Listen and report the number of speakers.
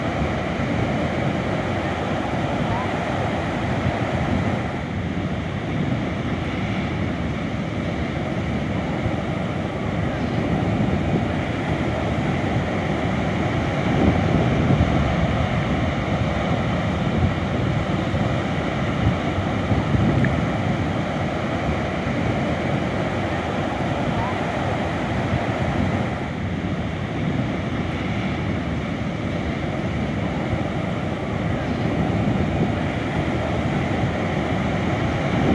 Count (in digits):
0